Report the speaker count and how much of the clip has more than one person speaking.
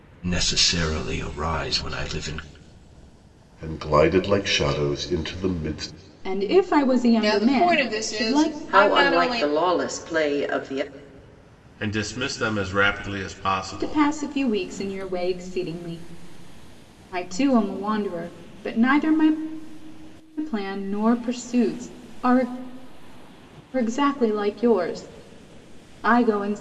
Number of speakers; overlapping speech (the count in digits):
6, about 10%